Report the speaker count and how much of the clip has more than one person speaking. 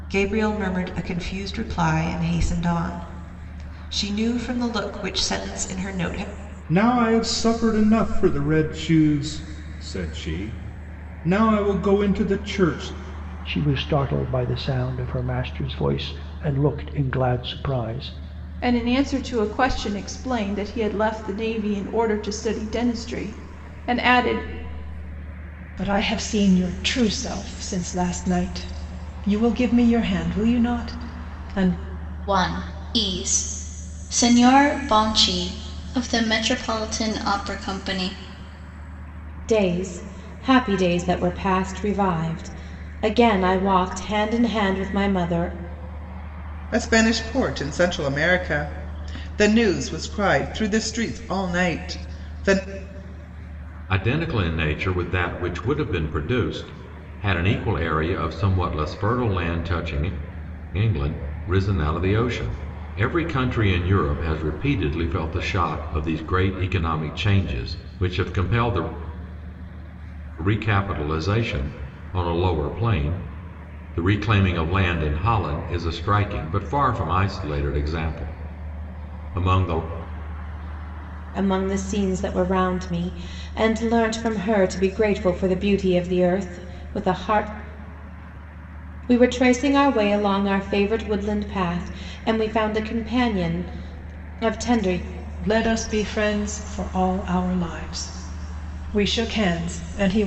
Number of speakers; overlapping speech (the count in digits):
9, no overlap